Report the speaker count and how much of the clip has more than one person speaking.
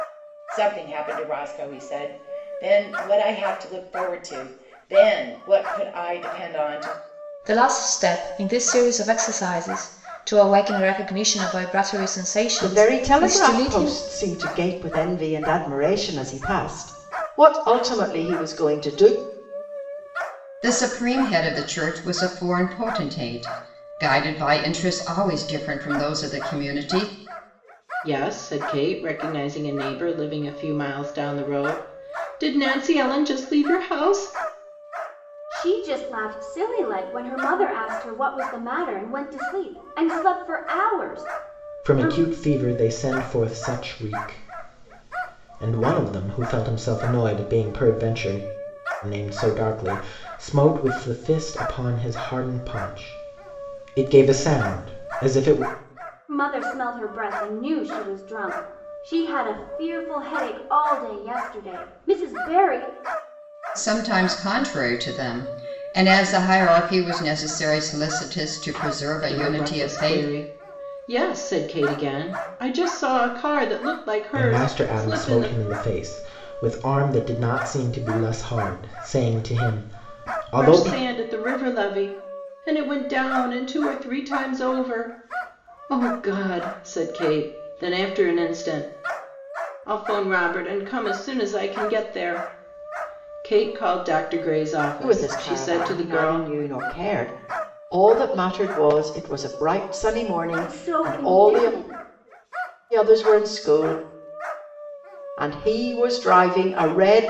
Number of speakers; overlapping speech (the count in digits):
7, about 7%